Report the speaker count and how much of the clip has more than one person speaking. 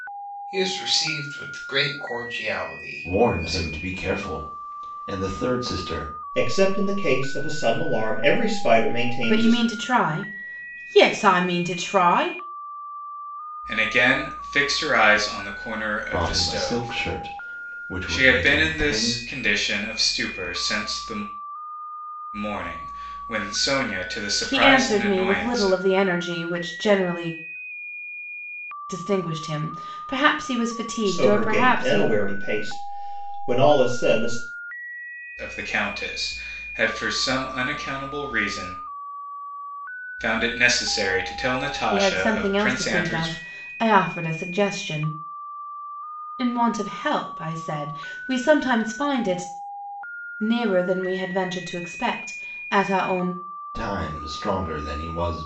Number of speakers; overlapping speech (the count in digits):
5, about 13%